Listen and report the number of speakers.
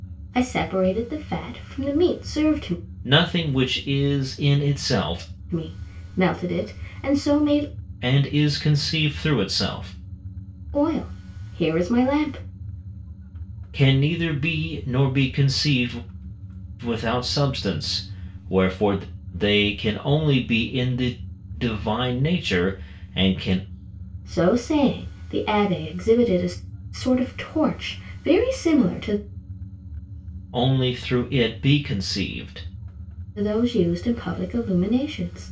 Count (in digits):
2